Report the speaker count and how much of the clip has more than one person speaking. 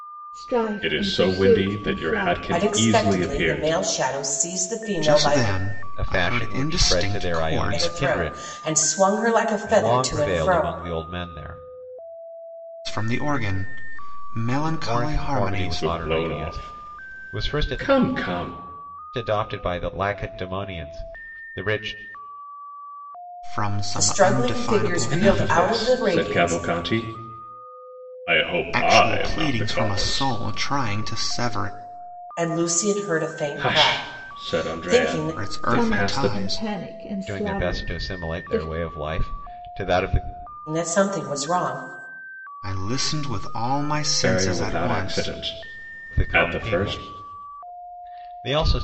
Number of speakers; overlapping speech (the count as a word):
five, about 43%